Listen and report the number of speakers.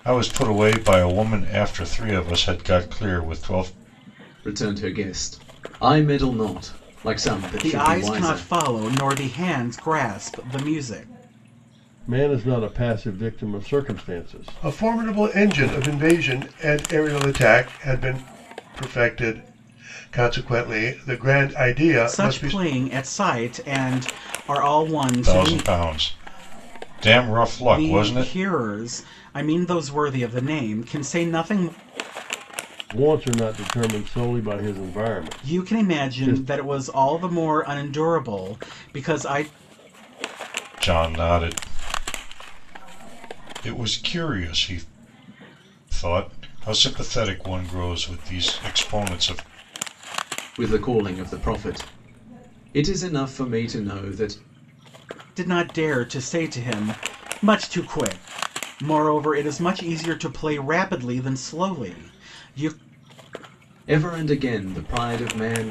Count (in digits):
5